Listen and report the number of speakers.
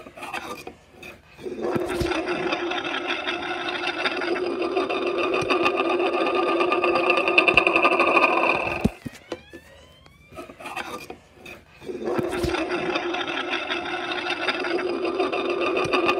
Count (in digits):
0